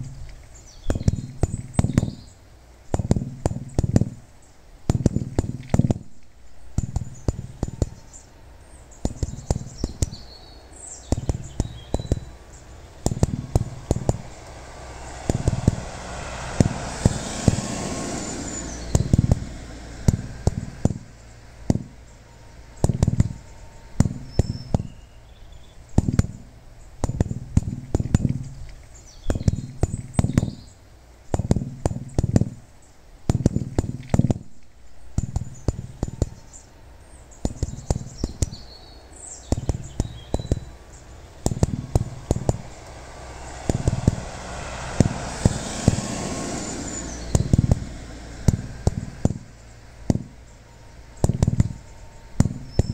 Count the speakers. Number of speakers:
zero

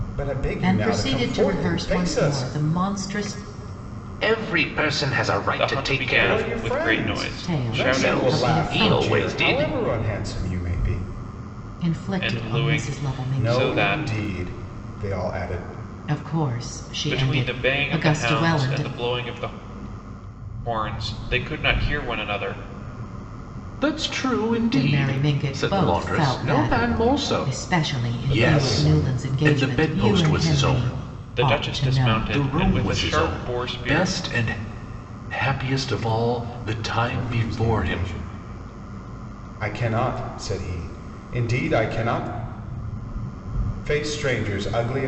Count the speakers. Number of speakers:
four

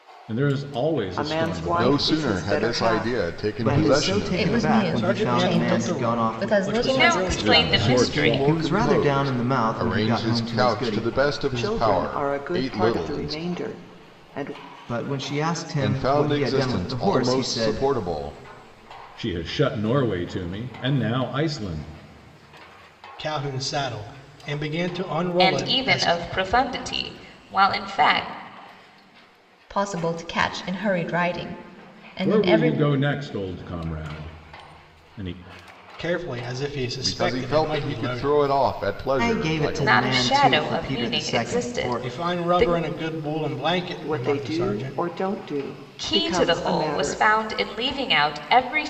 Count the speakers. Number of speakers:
seven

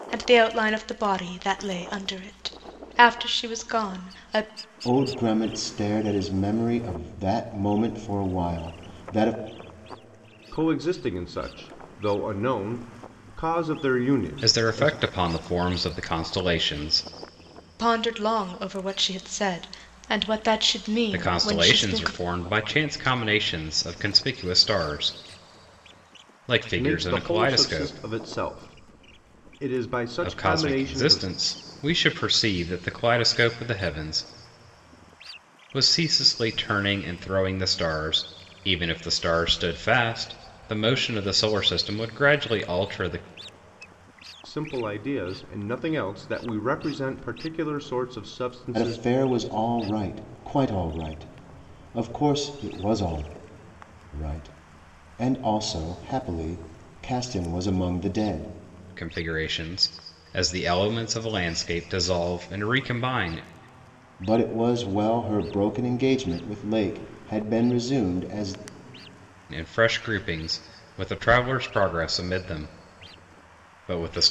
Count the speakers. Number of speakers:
four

